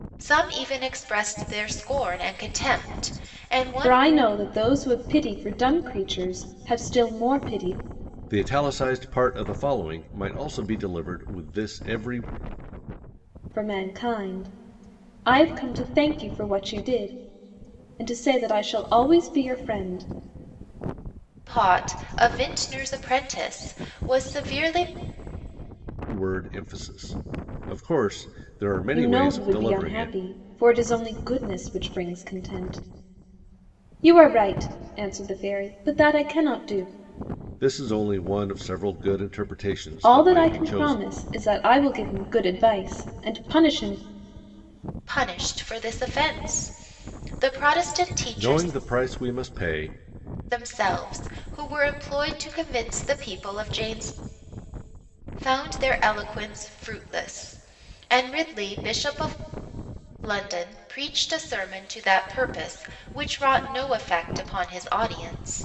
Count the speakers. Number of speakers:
3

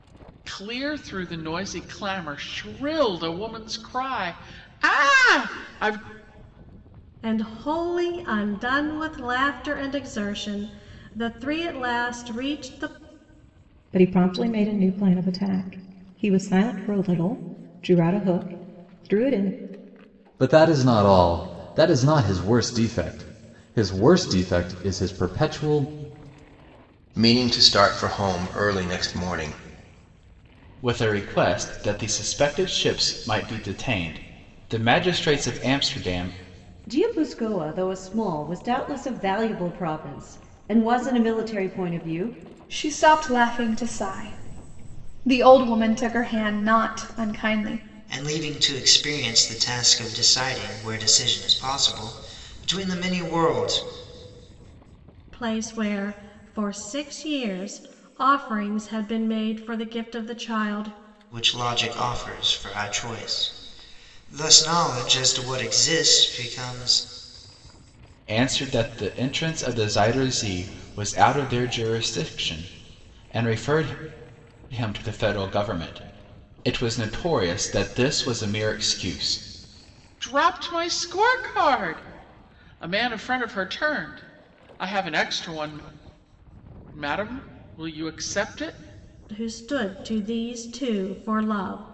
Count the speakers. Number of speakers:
9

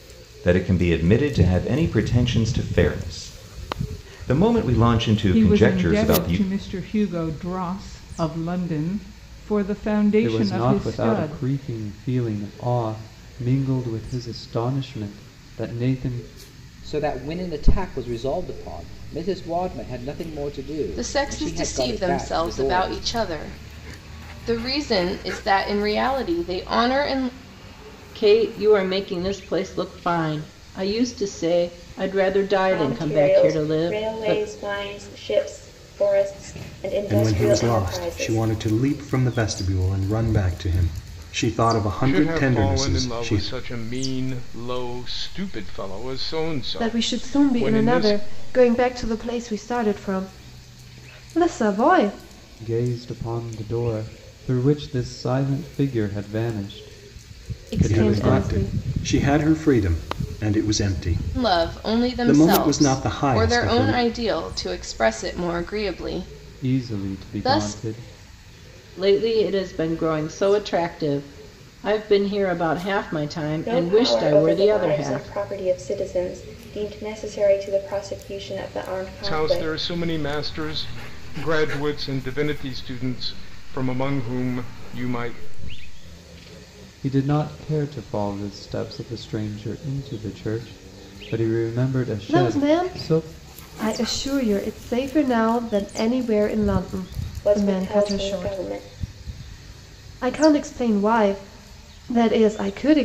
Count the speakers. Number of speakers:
10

